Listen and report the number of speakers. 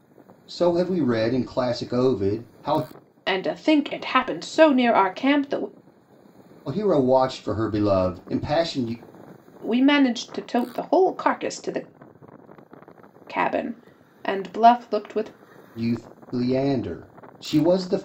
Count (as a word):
two